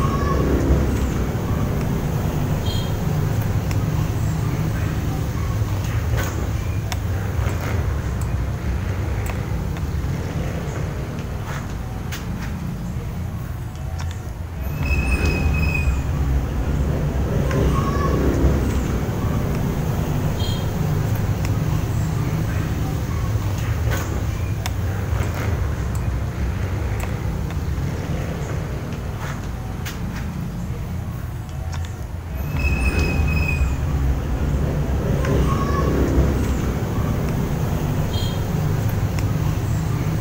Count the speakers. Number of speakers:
0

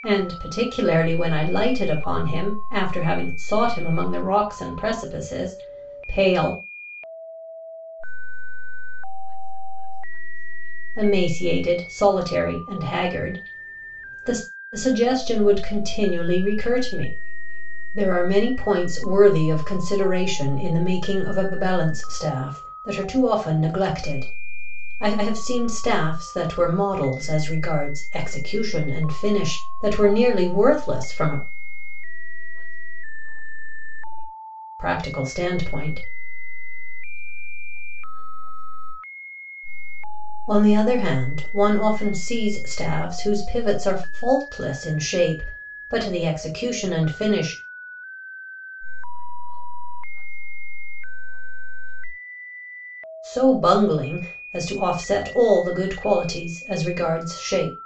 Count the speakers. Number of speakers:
2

